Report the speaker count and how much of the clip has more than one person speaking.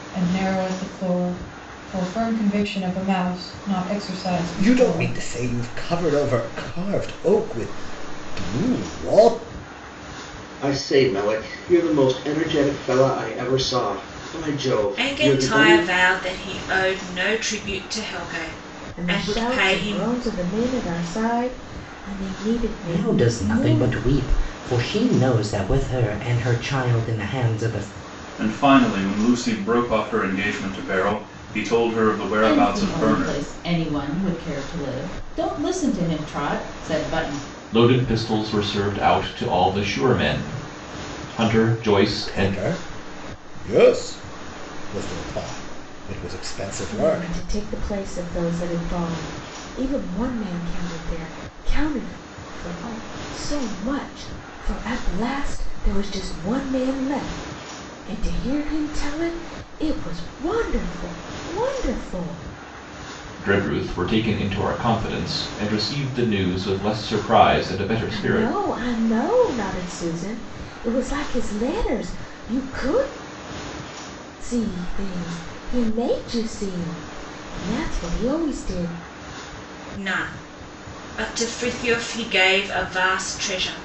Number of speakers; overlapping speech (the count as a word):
nine, about 7%